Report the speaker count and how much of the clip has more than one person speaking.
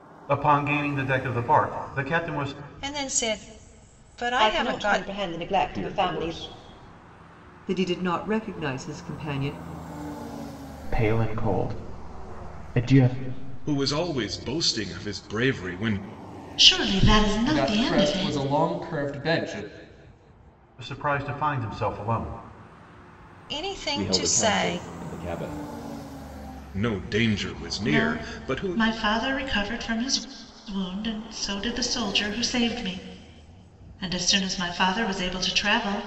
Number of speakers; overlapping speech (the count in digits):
9, about 12%